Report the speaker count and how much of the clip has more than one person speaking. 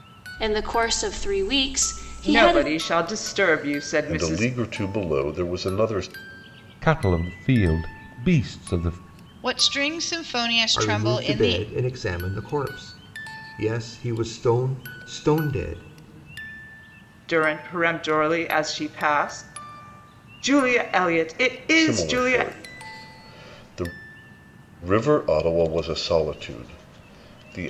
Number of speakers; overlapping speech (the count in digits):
6, about 9%